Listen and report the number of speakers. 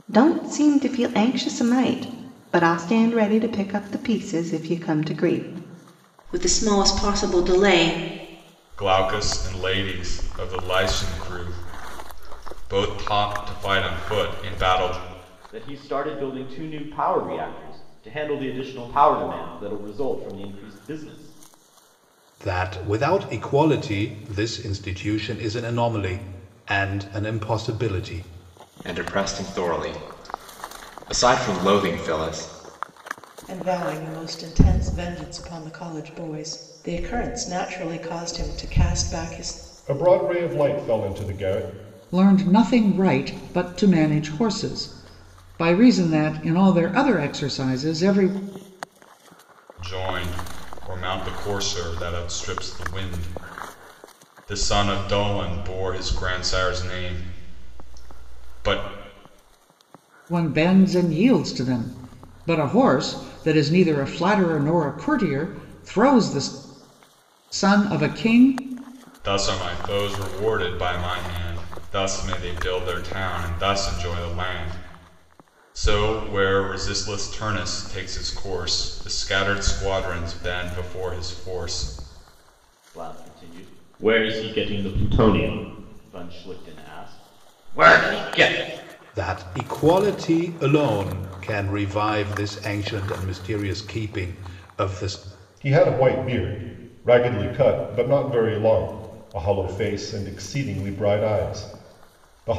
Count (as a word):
nine